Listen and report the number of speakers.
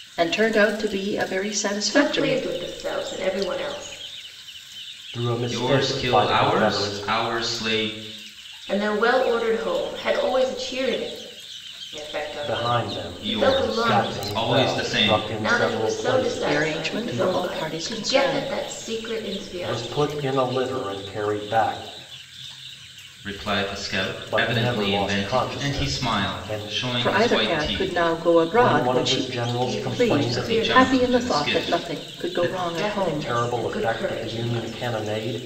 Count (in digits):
4